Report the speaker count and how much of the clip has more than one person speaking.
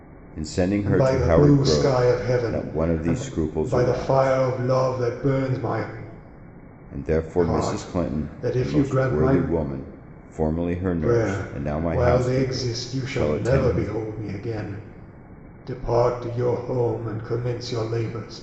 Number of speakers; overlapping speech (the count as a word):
two, about 45%